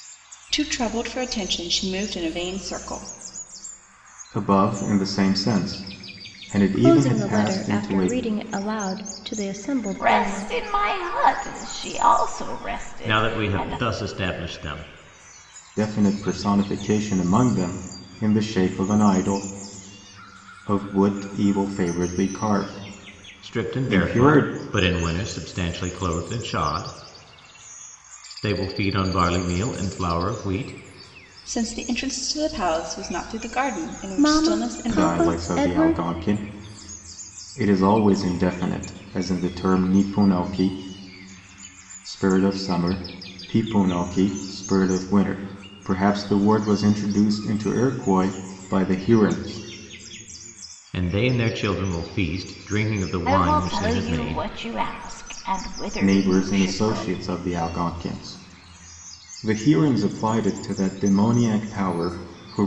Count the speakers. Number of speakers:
five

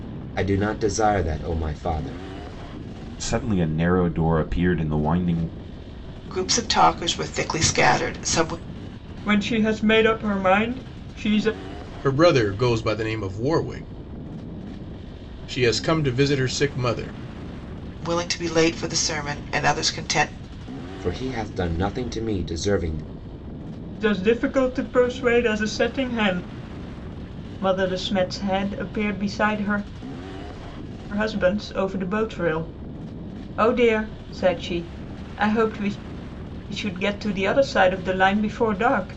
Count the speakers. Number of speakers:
five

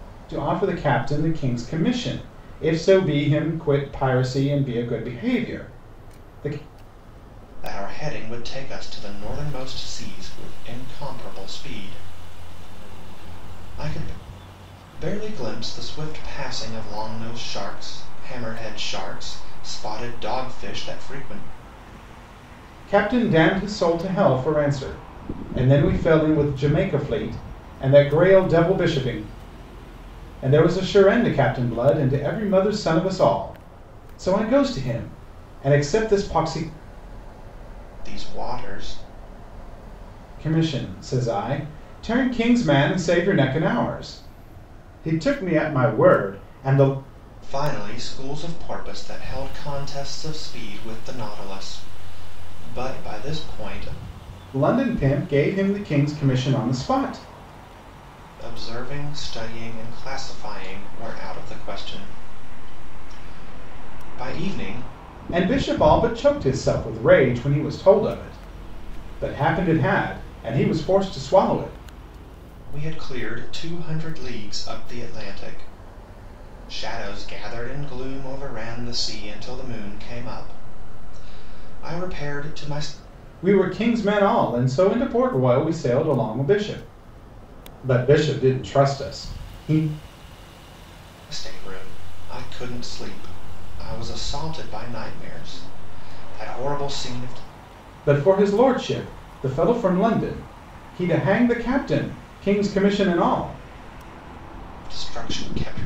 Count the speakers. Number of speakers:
two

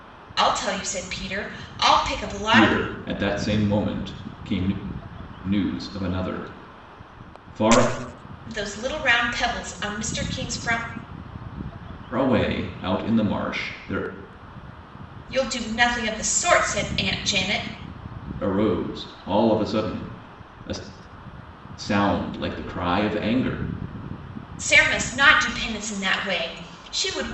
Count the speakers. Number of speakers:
two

